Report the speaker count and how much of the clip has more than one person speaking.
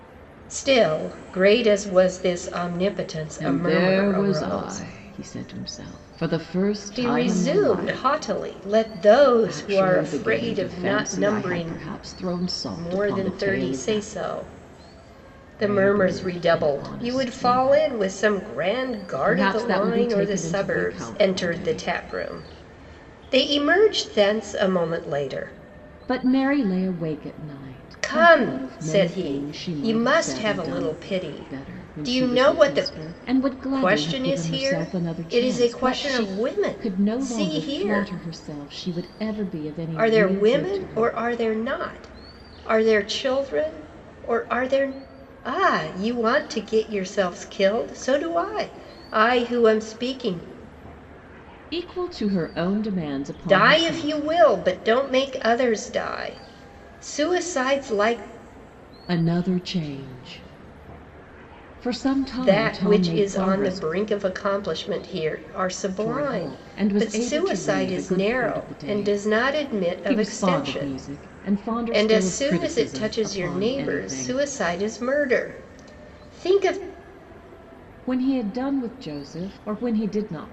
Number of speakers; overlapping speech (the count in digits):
2, about 38%